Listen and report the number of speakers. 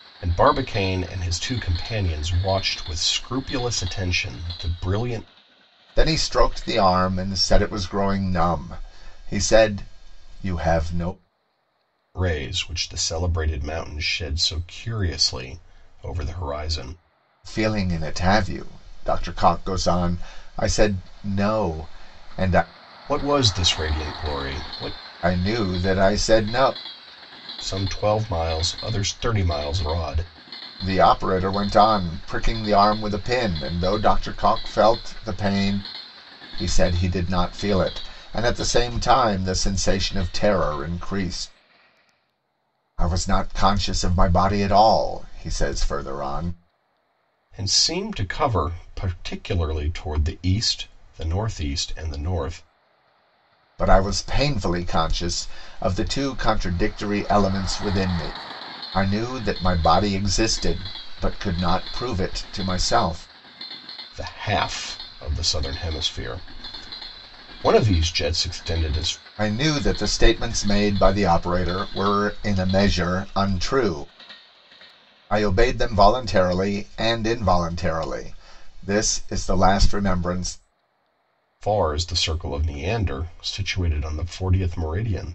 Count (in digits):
2